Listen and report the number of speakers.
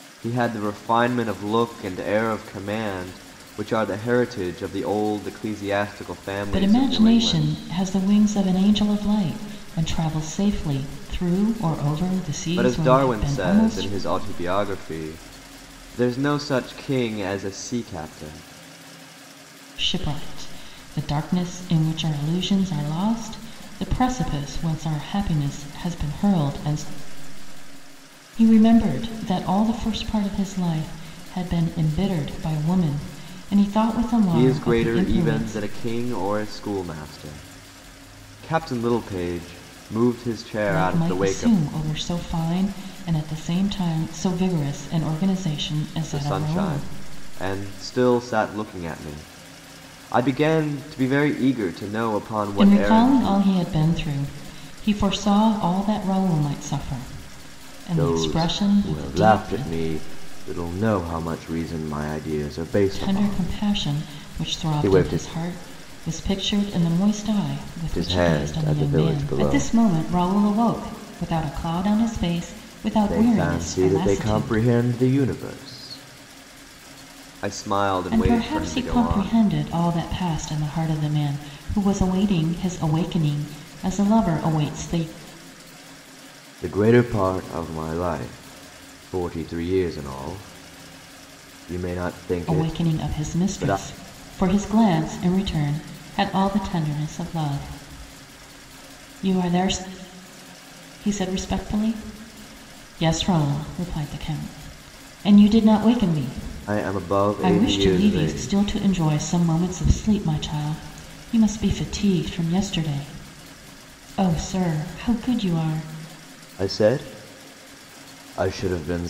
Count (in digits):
2